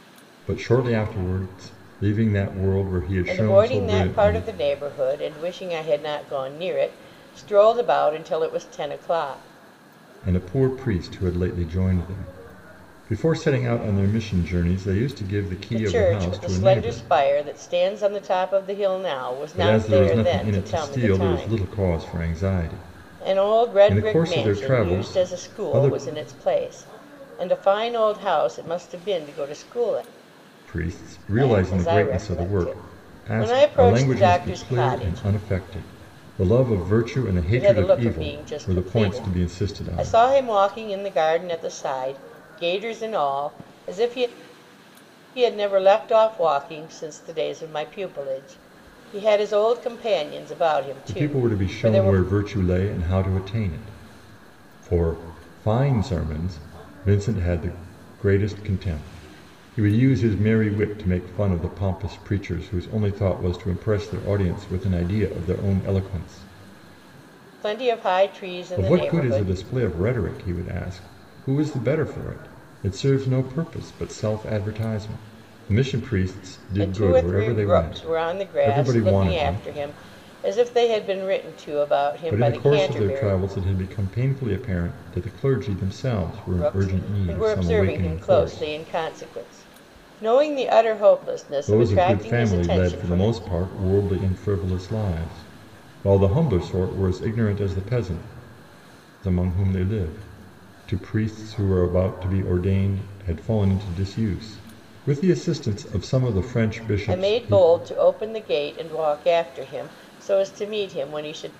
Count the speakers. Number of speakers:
two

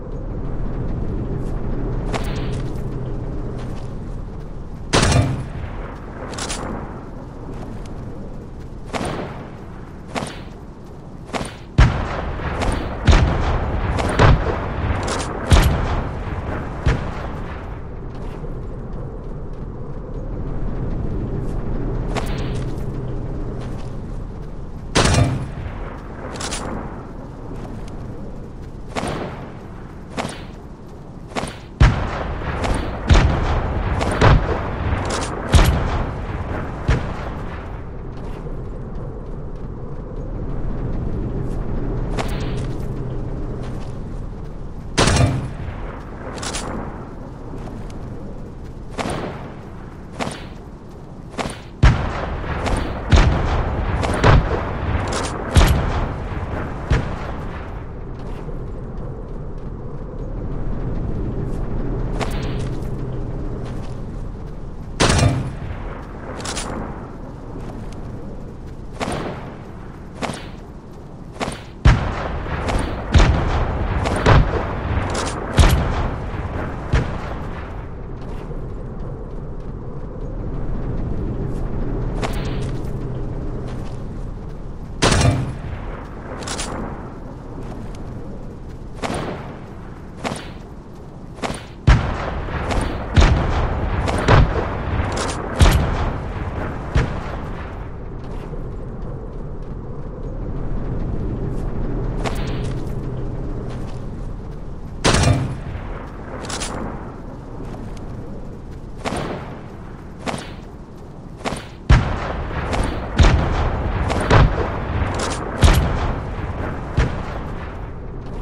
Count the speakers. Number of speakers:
zero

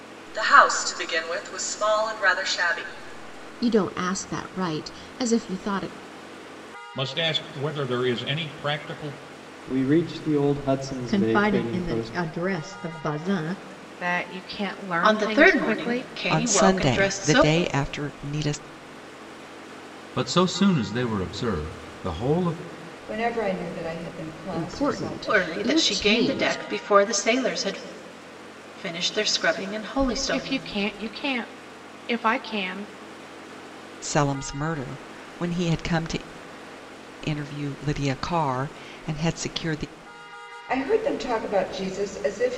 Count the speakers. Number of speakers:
ten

